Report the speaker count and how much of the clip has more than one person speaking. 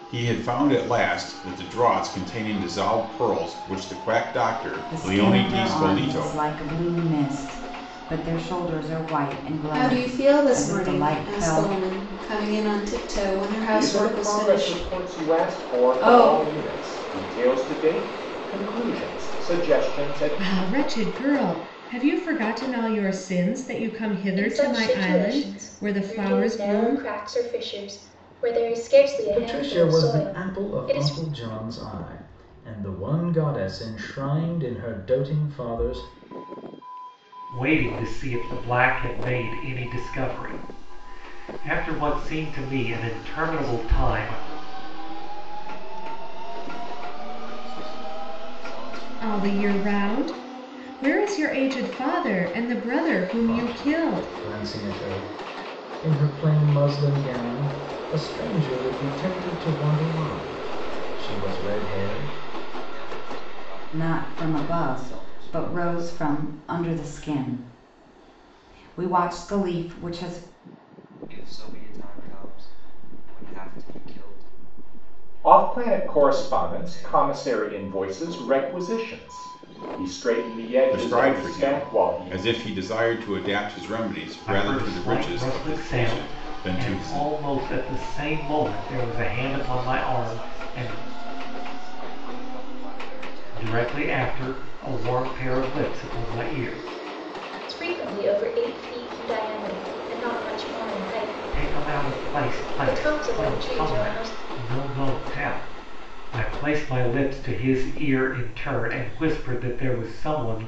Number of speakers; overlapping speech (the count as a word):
nine, about 30%